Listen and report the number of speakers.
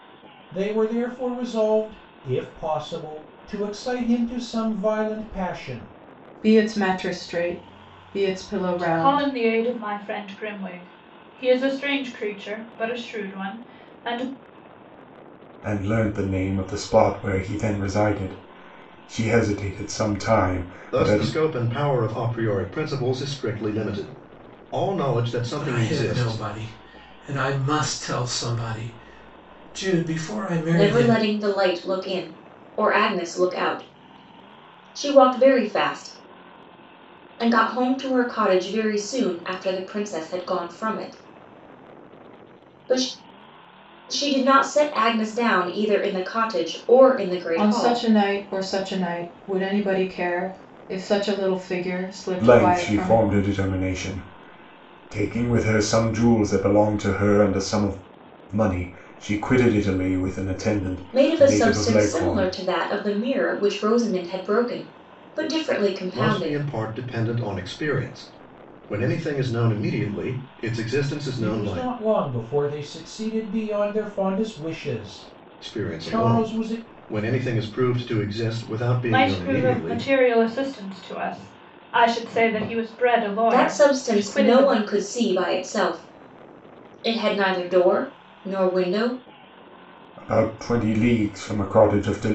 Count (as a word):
seven